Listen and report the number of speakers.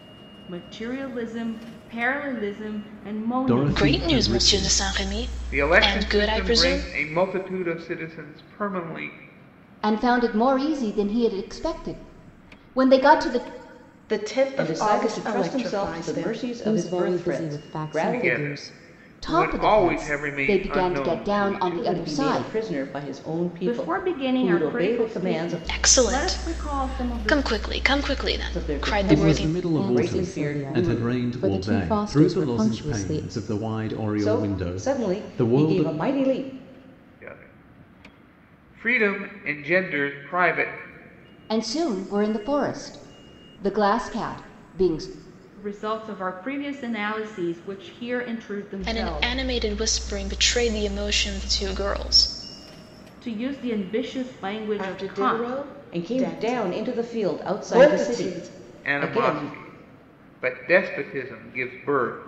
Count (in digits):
8